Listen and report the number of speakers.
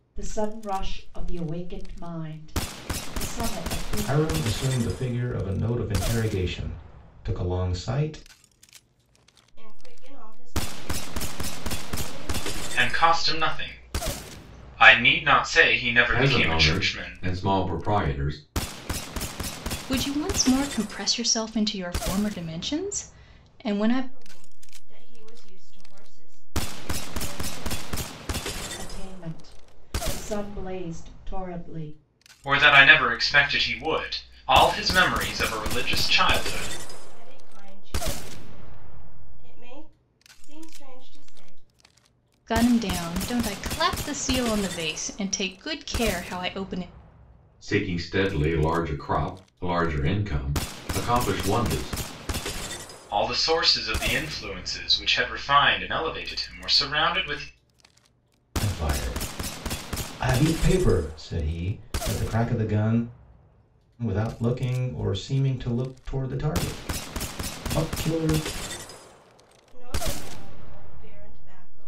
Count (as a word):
six